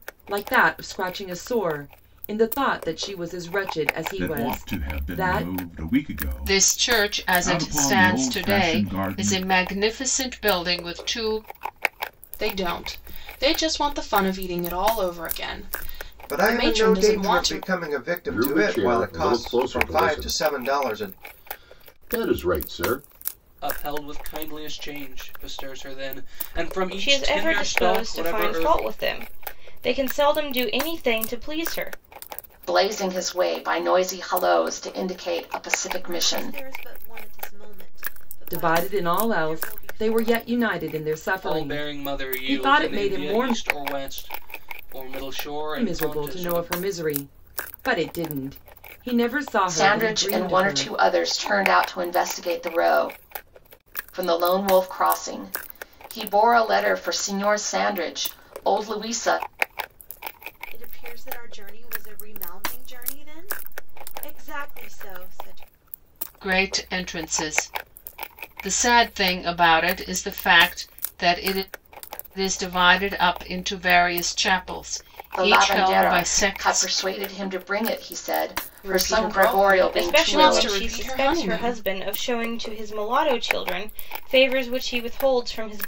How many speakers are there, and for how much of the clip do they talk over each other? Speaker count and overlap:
10, about 26%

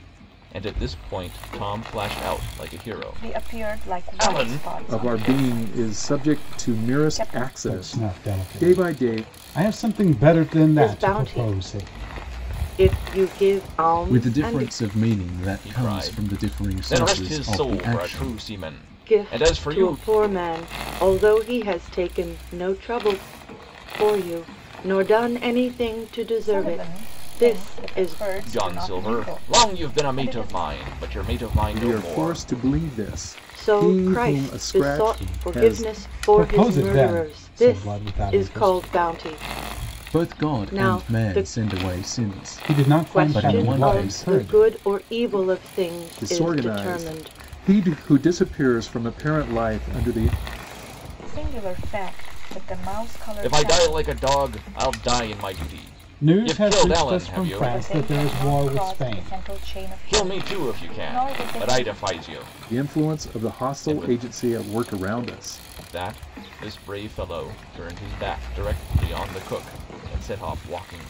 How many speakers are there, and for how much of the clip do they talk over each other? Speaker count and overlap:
6, about 47%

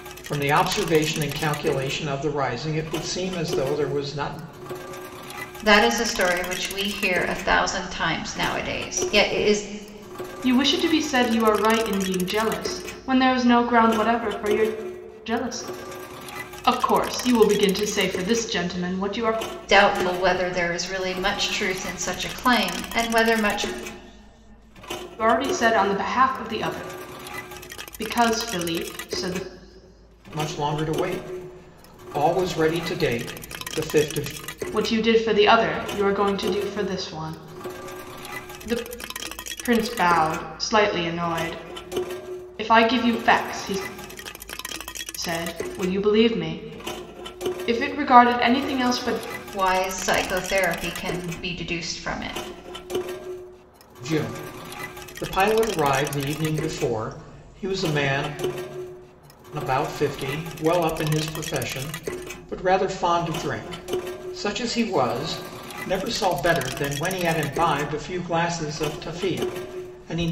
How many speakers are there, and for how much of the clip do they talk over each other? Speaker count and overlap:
3, no overlap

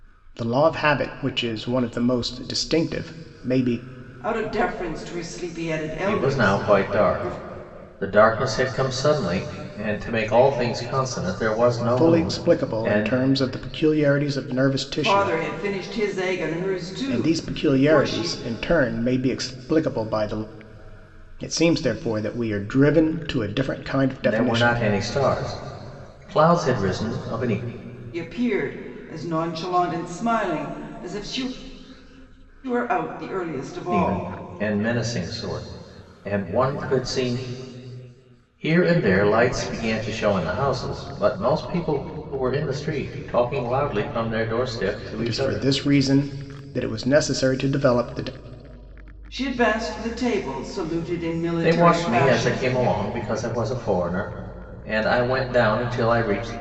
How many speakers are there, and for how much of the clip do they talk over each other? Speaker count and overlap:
3, about 12%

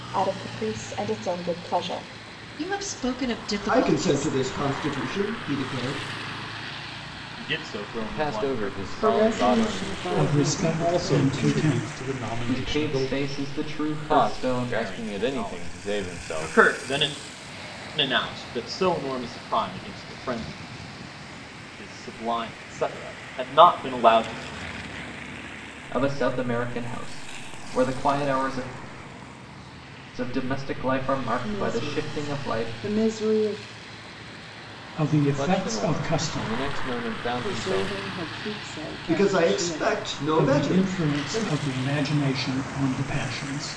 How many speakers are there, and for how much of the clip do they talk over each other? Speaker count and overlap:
9, about 31%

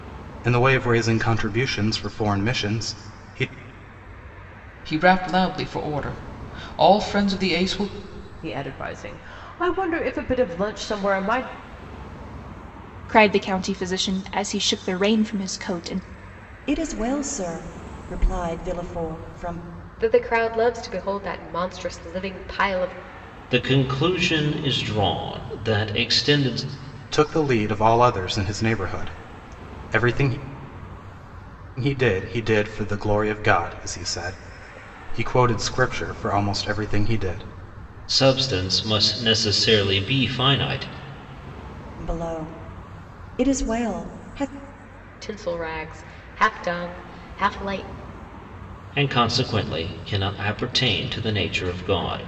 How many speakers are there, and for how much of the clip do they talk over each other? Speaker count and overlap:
7, no overlap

